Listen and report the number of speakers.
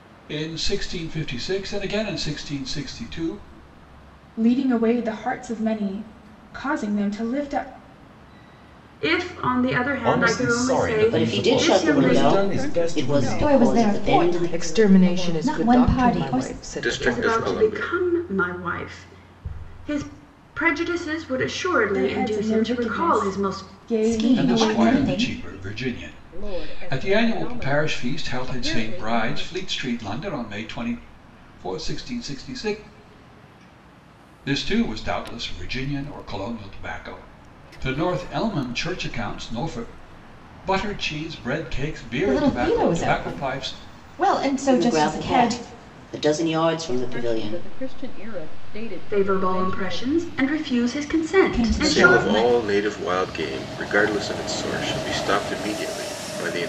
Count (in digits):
9